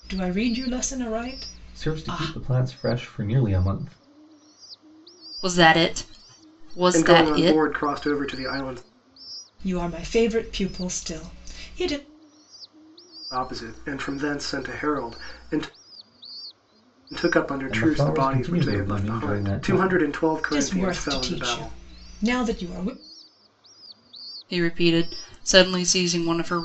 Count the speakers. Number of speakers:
4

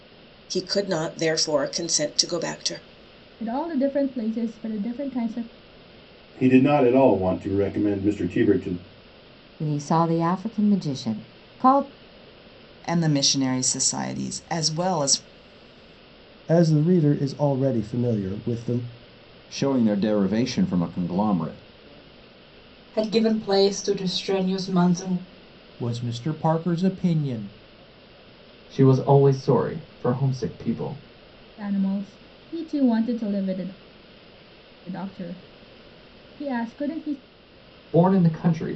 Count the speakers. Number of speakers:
10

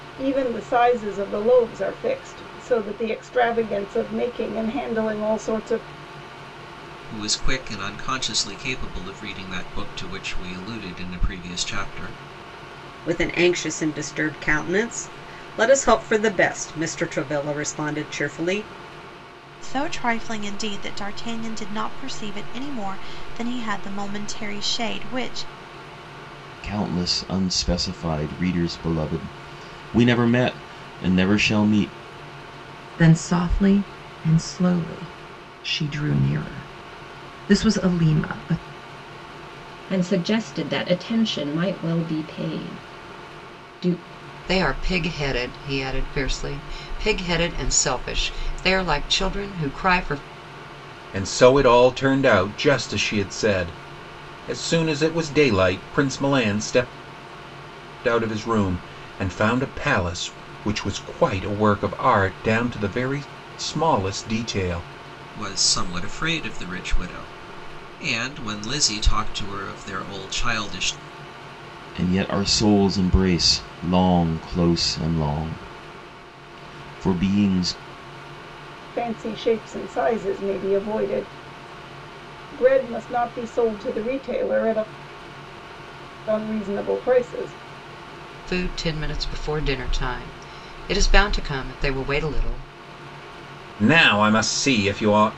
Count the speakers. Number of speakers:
9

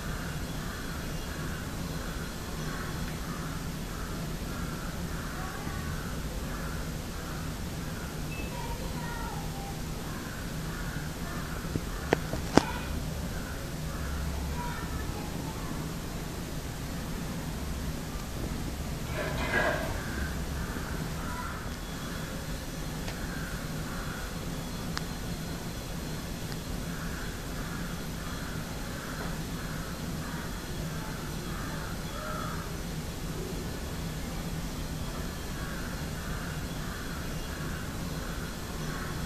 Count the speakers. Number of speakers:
0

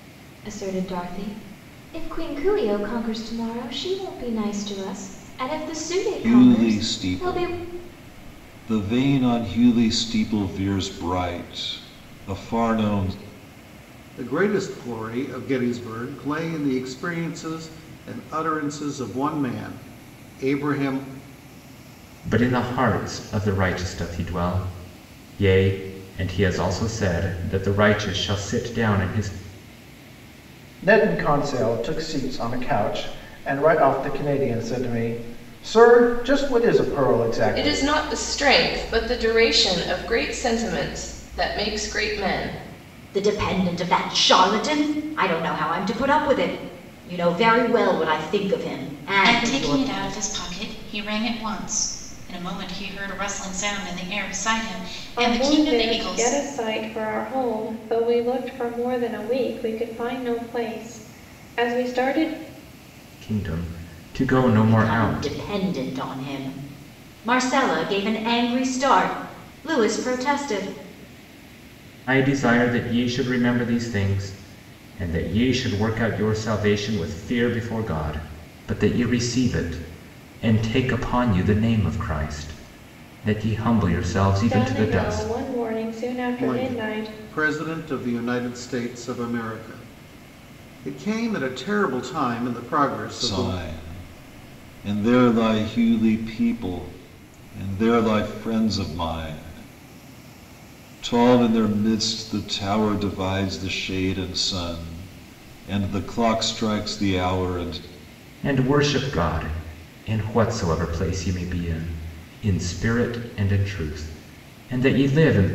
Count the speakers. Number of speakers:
9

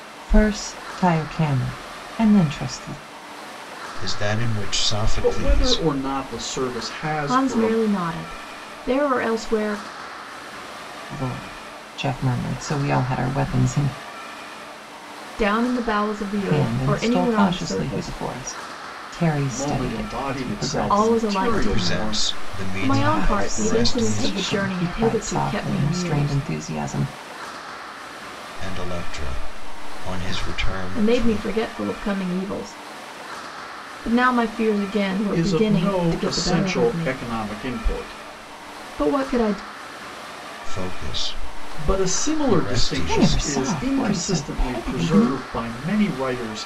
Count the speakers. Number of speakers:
4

